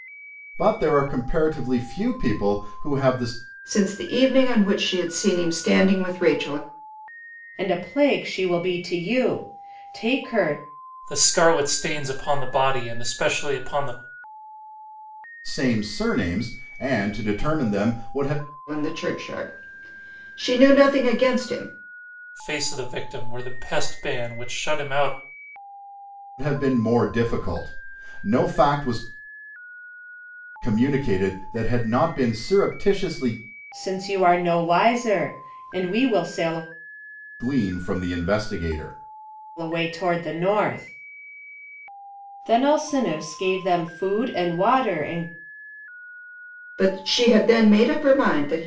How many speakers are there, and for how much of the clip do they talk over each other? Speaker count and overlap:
4, no overlap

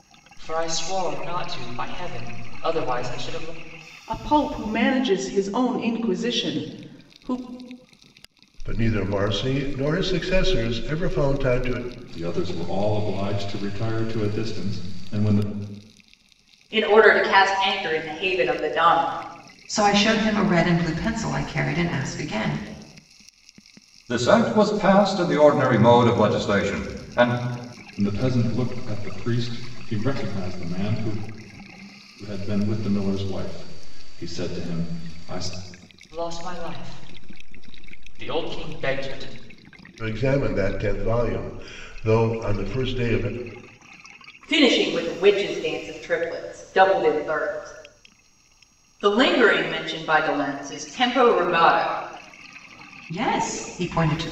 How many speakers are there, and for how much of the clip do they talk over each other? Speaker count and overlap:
7, no overlap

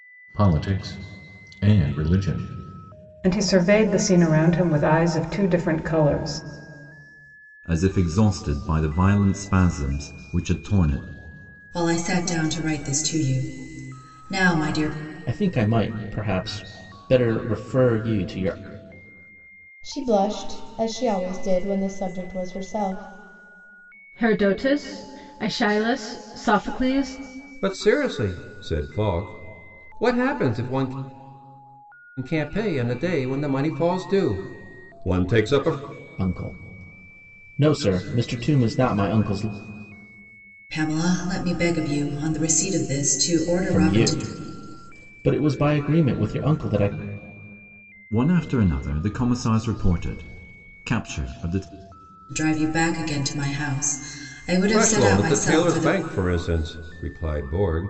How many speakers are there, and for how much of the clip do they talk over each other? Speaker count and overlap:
8, about 3%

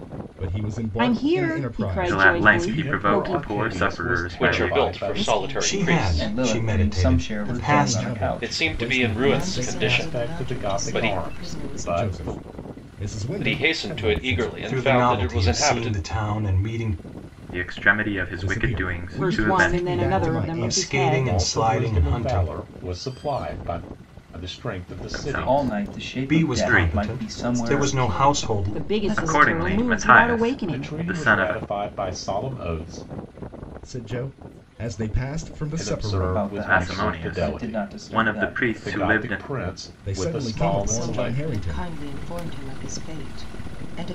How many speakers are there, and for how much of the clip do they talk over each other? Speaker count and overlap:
8, about 68%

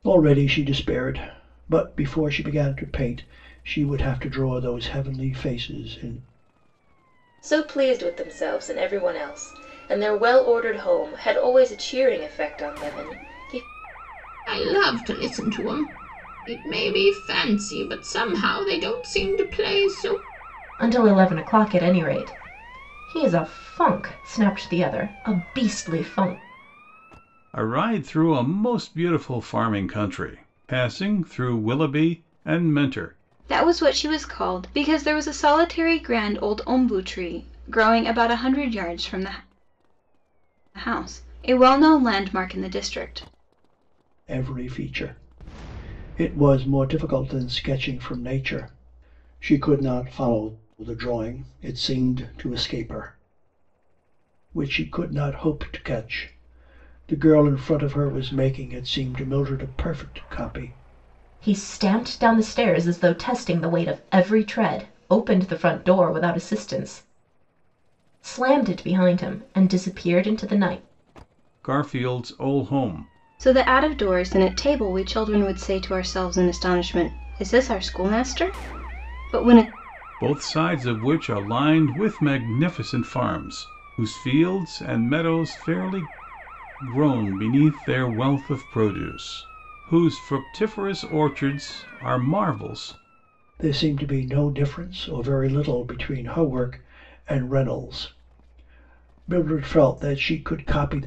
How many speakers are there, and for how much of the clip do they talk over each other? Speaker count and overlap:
6, no overlap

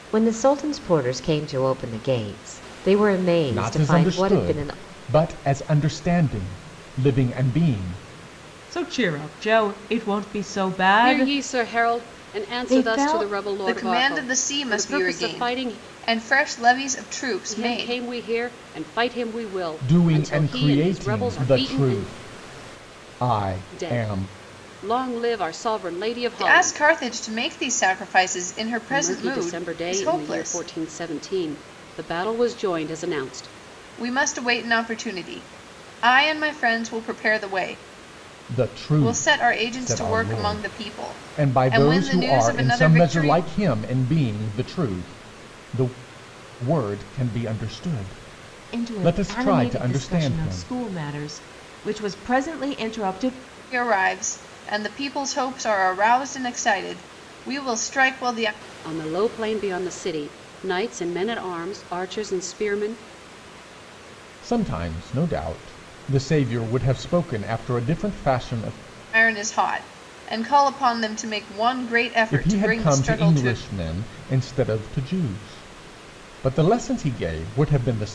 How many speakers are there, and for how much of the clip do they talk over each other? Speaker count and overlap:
5, about 24%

